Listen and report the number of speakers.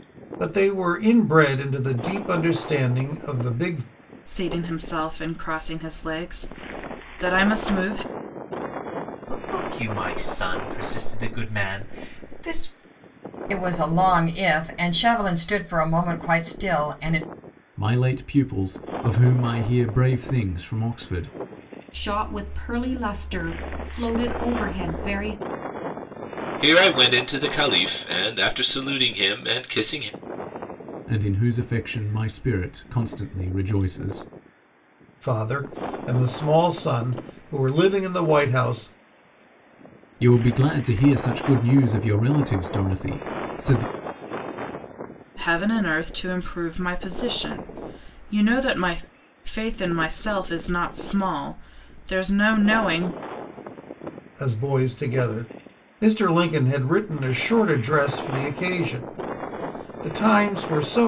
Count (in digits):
7